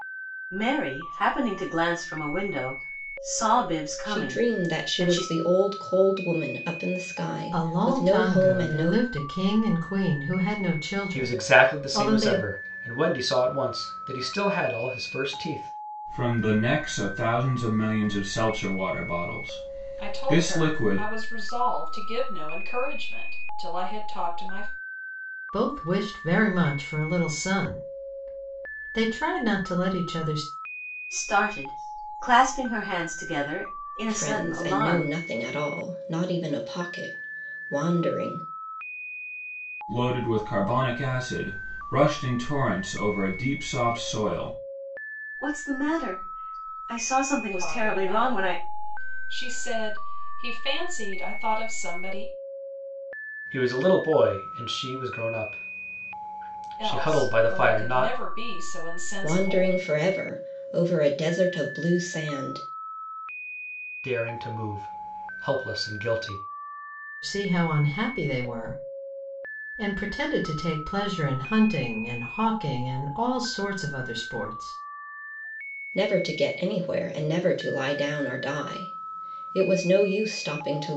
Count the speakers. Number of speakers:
6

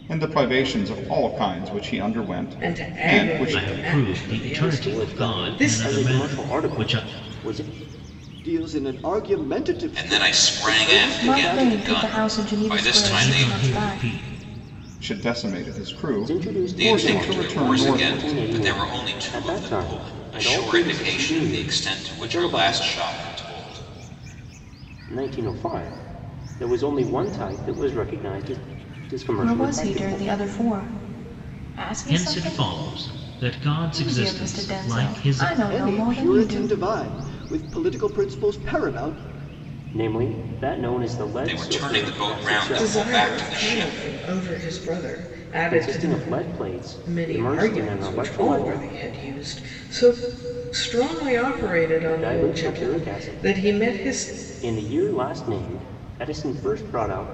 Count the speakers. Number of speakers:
7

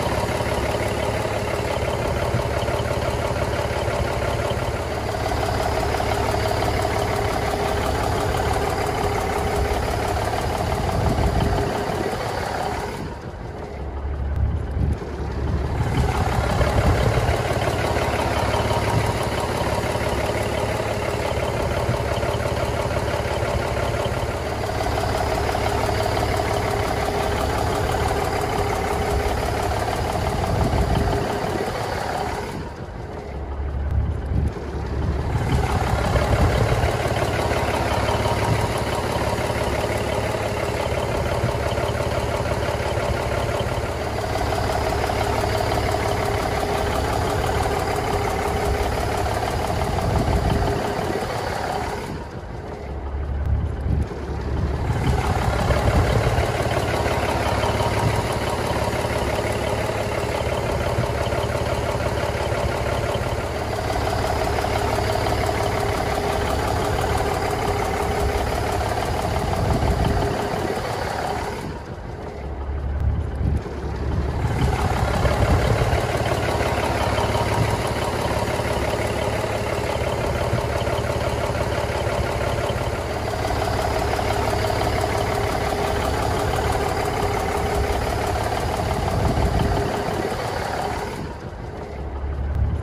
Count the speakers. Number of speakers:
0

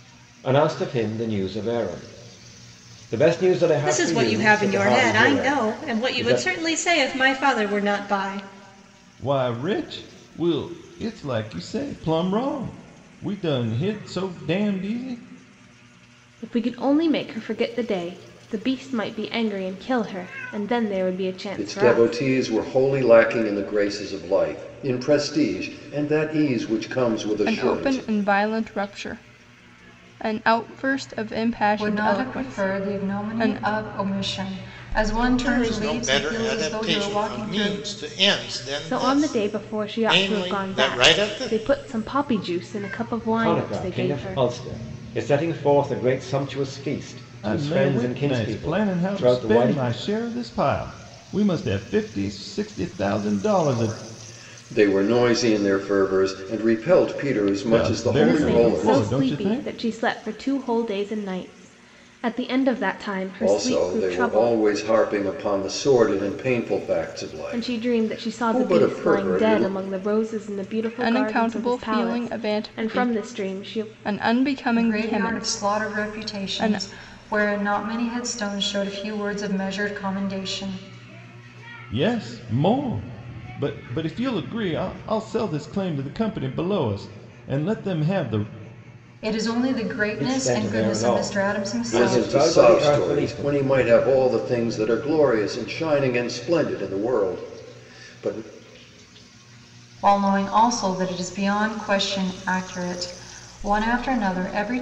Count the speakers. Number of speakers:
8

